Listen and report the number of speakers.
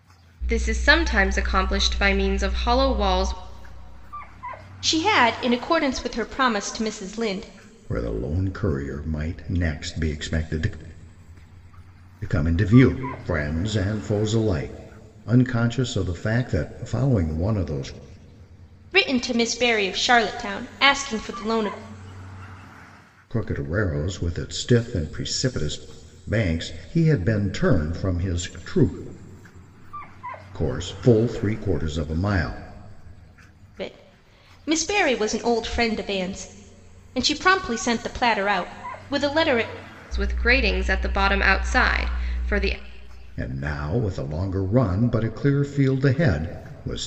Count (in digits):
3